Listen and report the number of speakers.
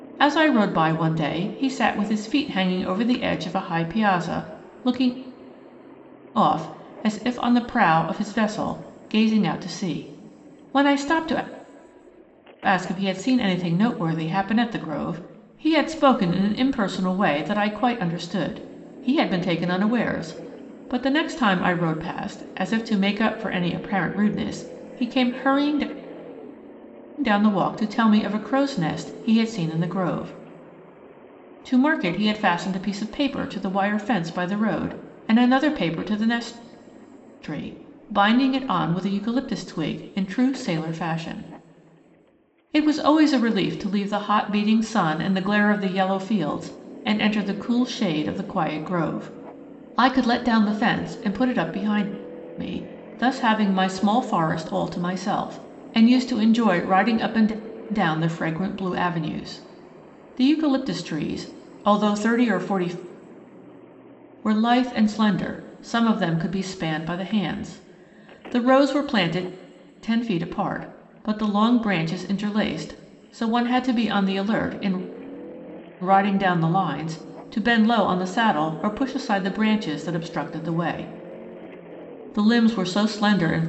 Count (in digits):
1